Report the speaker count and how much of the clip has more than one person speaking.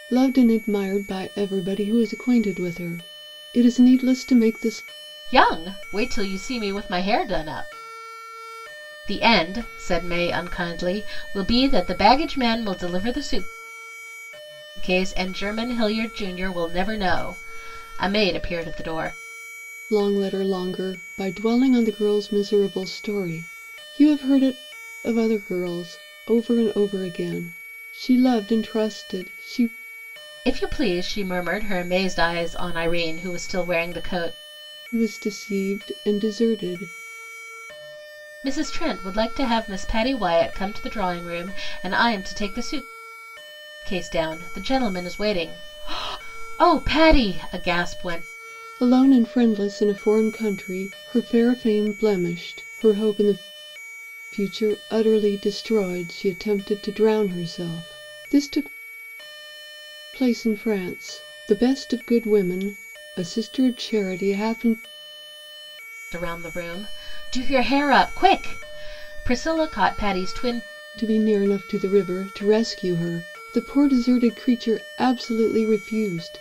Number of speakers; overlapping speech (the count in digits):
2, no overlap